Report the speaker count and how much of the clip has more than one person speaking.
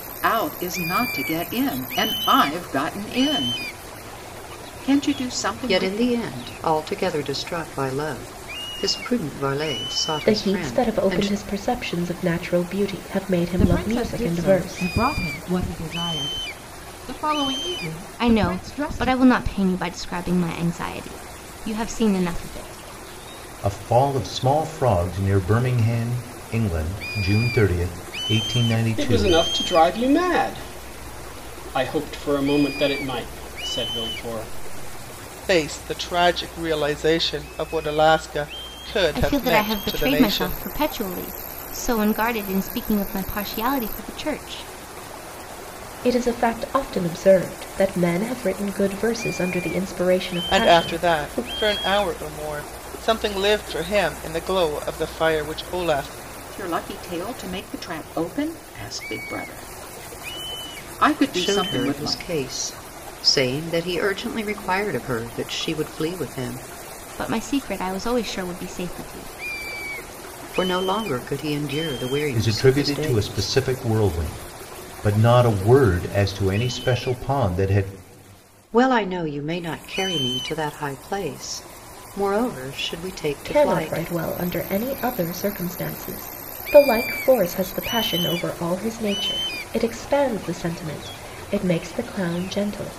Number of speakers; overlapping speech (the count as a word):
eight, about 10%